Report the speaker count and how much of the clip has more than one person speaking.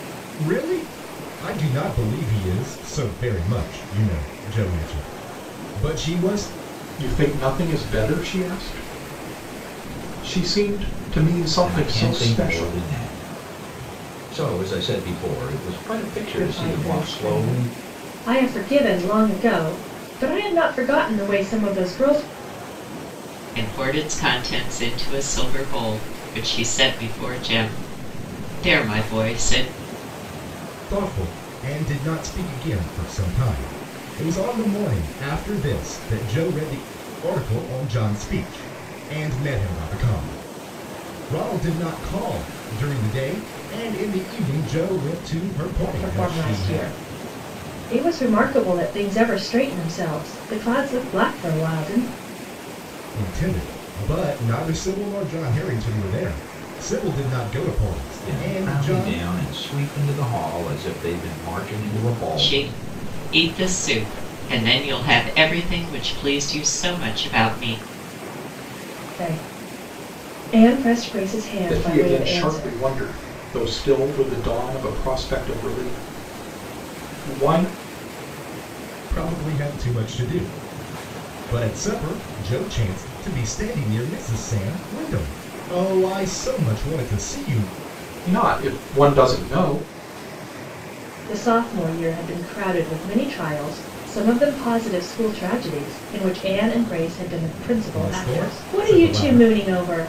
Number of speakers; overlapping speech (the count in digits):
5, about 8%